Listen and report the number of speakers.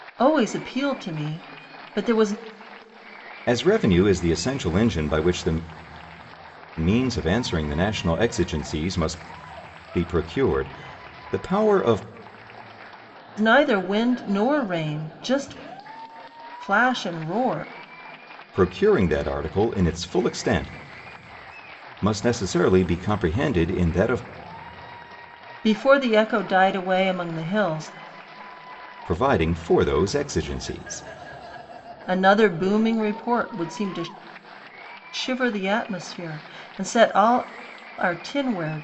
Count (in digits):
2